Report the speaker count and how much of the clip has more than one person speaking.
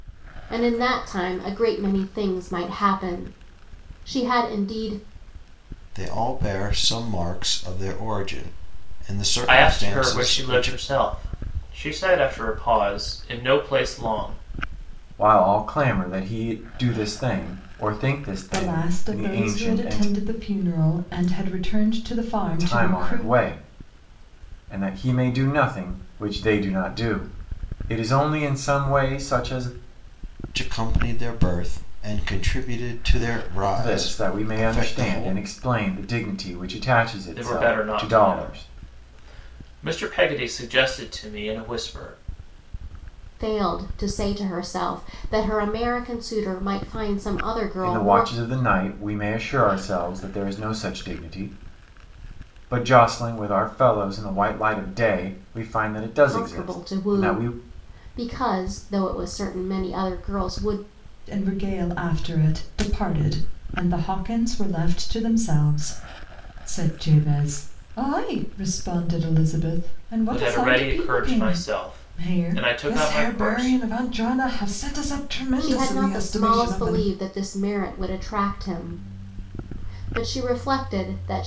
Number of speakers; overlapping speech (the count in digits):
5, about 16%